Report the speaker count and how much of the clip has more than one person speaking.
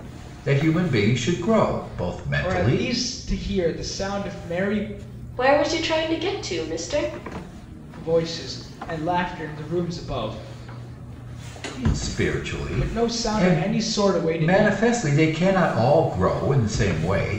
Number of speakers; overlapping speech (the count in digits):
3, about 10%